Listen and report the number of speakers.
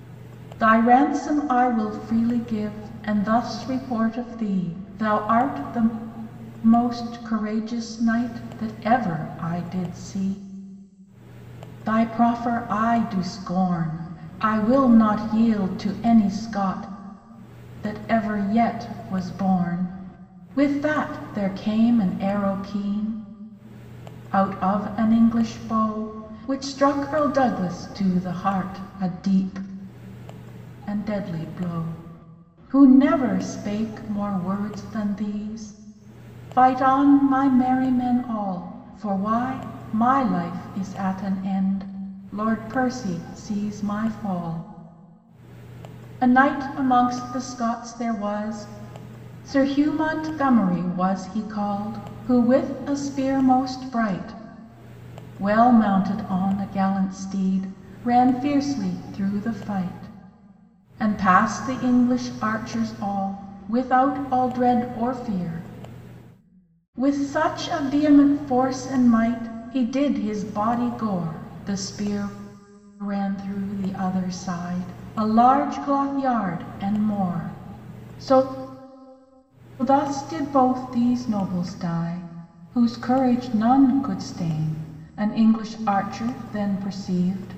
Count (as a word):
one